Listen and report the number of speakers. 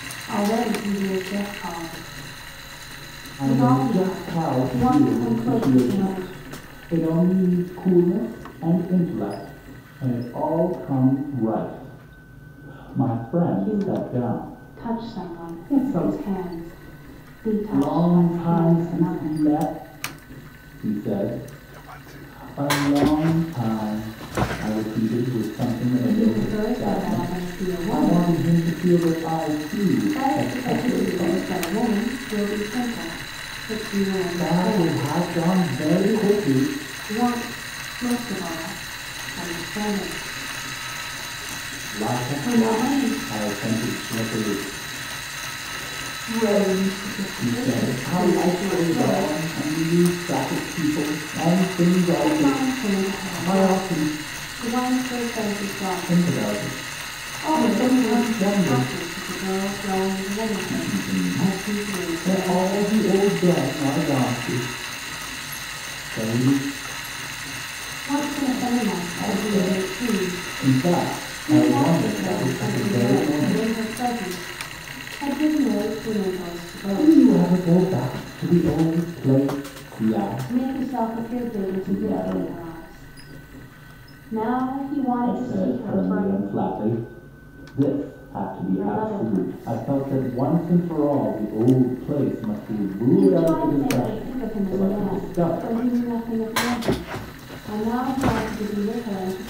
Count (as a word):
two